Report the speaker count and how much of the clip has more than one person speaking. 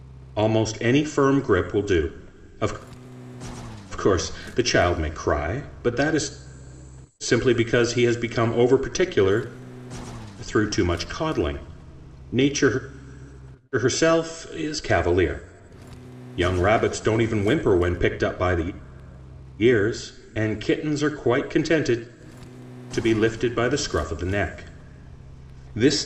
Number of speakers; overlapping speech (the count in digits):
1, no overlap